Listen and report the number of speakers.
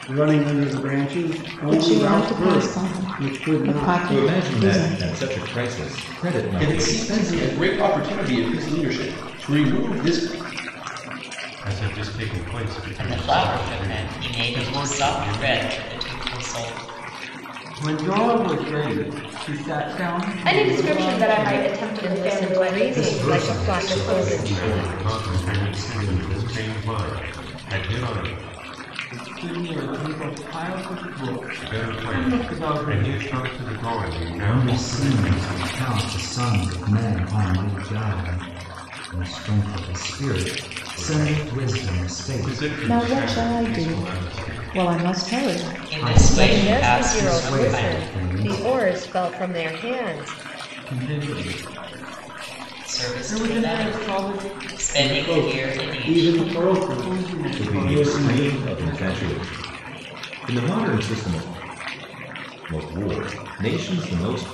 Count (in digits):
10